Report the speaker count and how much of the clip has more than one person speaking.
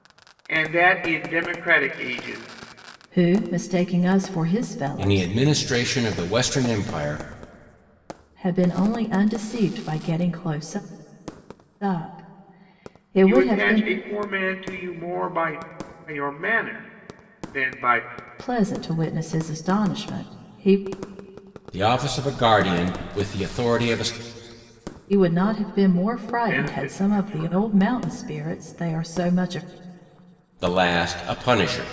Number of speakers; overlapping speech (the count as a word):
three, about 8%